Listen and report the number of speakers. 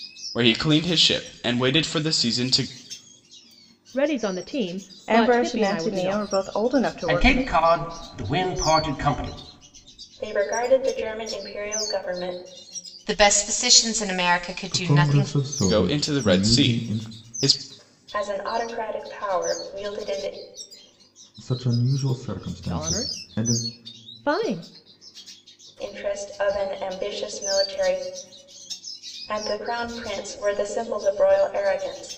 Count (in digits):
7